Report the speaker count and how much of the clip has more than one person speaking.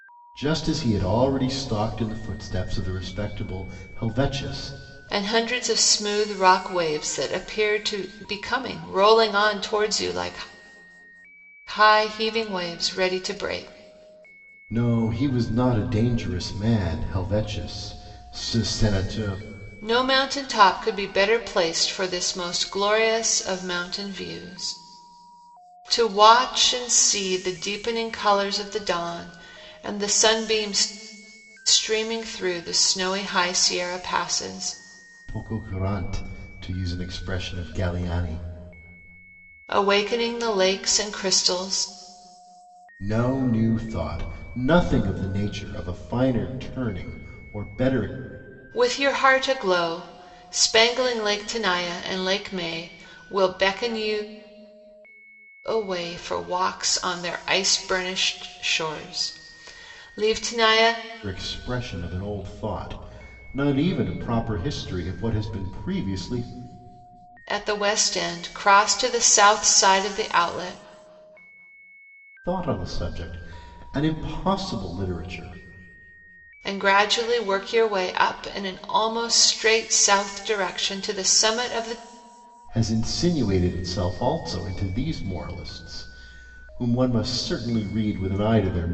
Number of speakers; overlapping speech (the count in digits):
2, no overlap